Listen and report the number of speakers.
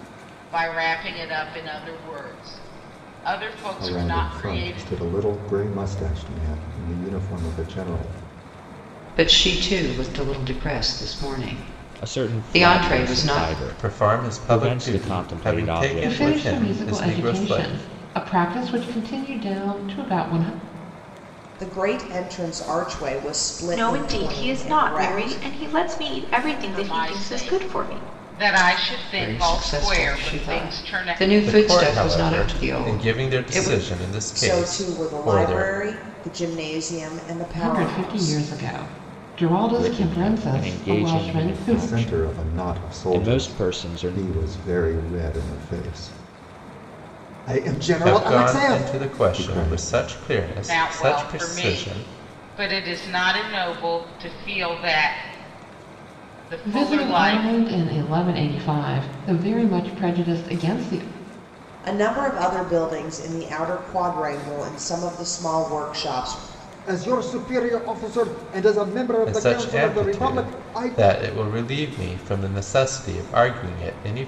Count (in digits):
8